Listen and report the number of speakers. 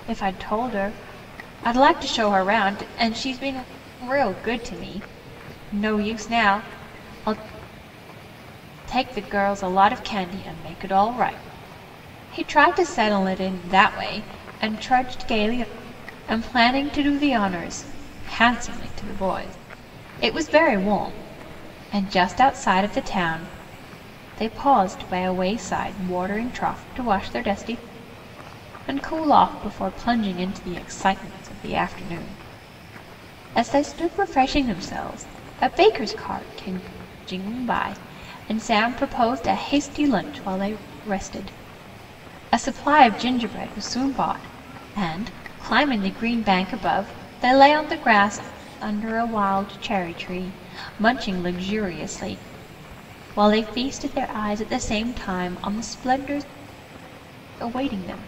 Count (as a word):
one